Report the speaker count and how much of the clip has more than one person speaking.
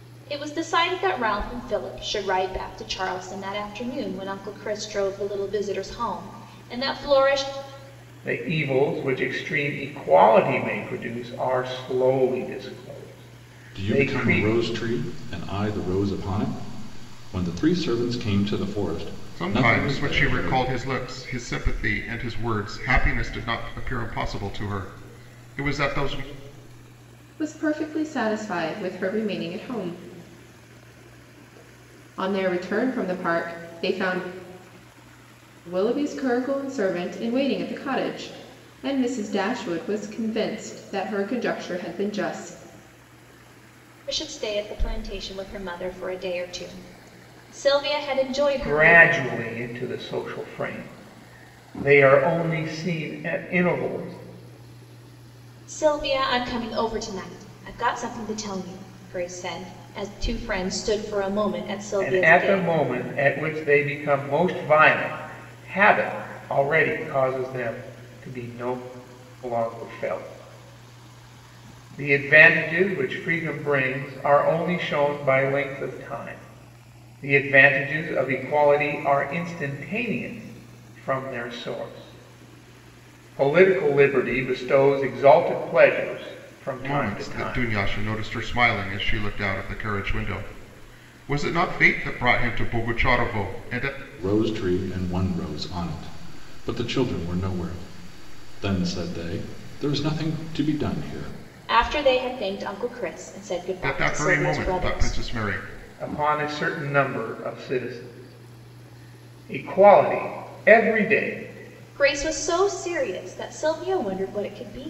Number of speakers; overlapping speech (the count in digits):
5, about 5%